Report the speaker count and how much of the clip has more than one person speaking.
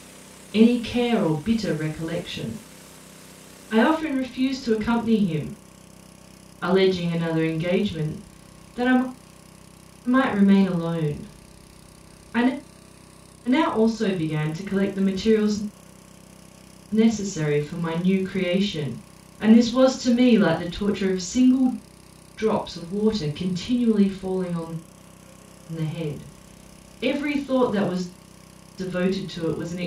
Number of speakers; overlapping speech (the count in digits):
1, no overlap